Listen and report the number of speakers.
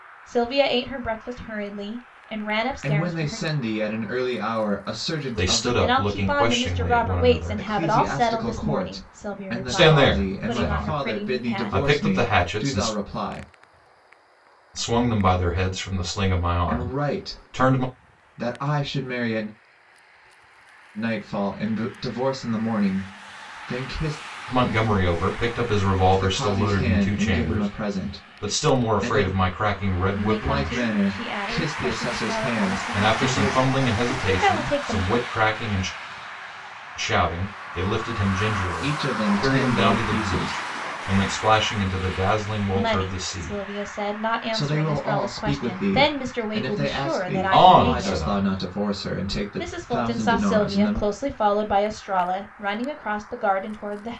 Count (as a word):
three